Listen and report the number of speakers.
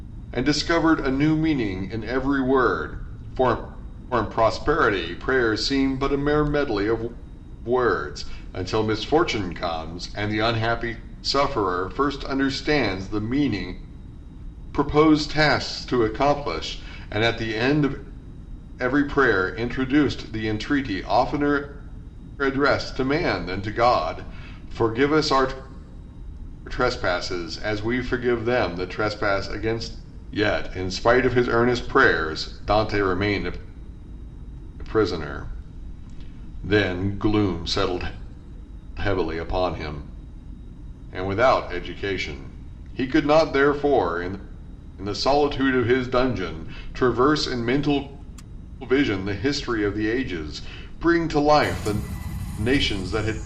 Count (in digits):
1